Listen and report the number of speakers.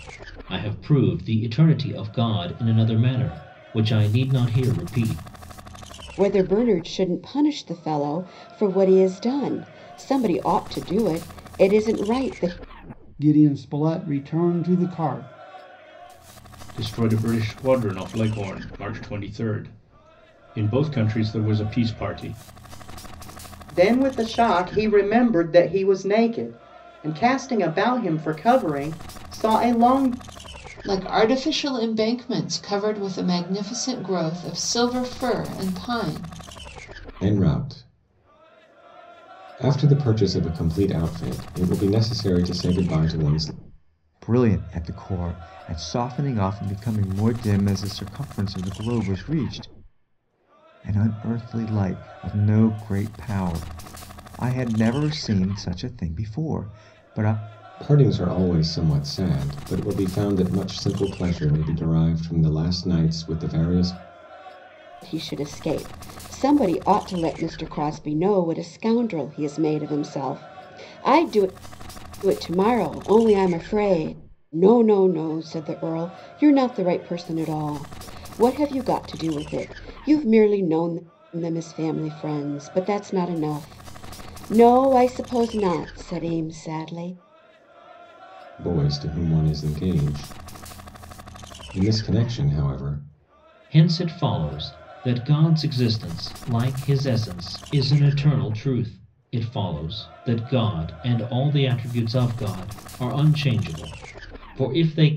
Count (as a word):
eight